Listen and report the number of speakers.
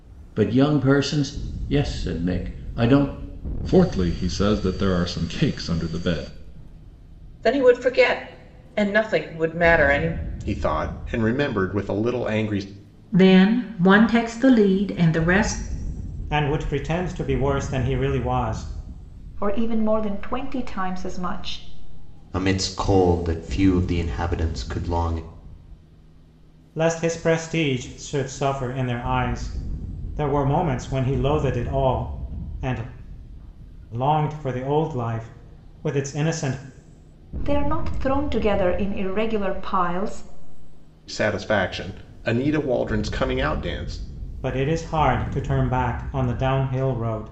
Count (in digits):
8